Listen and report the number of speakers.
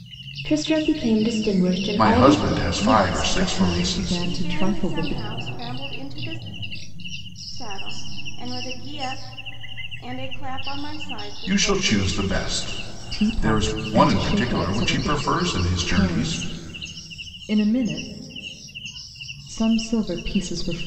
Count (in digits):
4